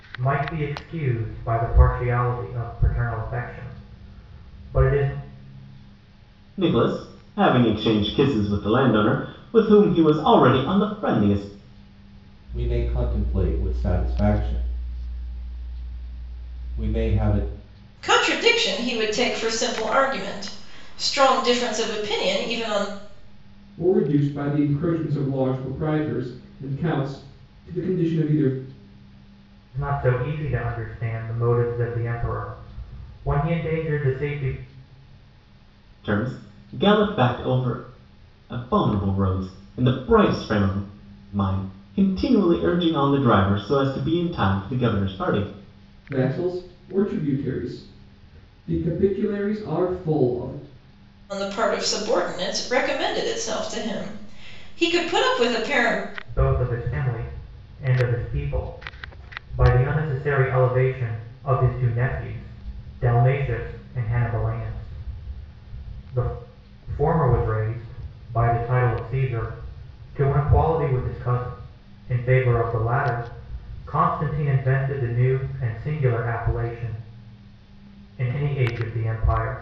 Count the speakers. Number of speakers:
5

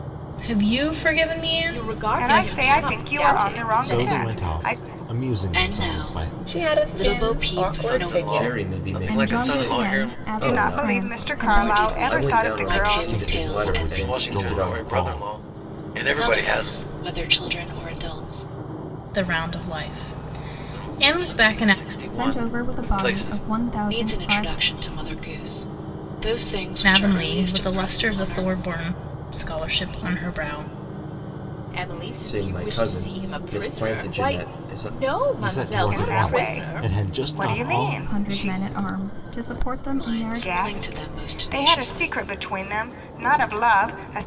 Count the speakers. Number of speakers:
9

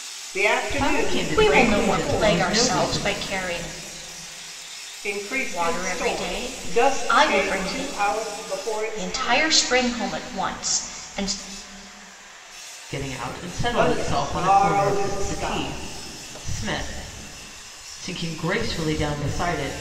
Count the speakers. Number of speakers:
3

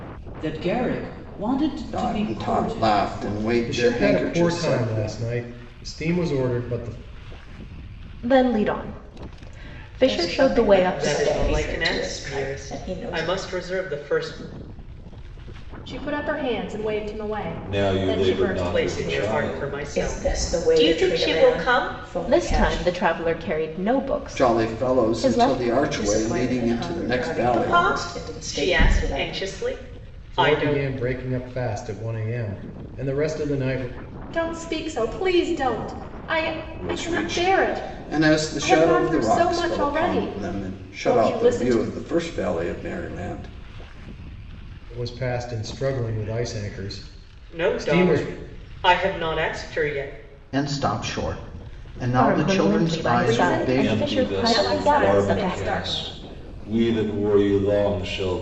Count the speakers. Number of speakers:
8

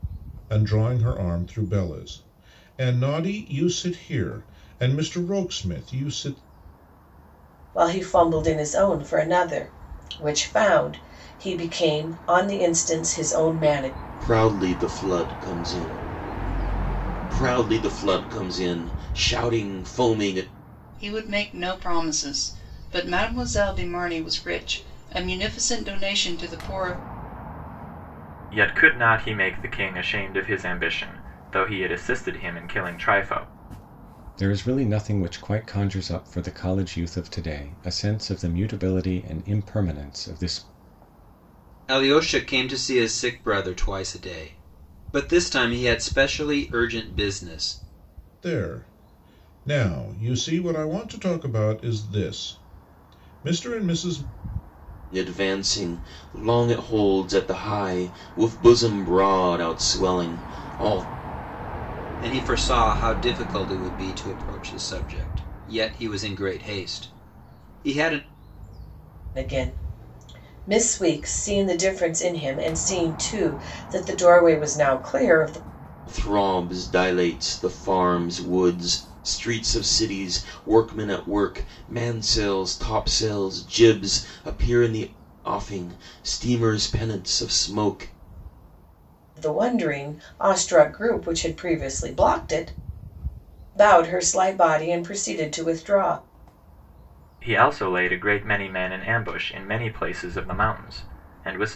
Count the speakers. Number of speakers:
7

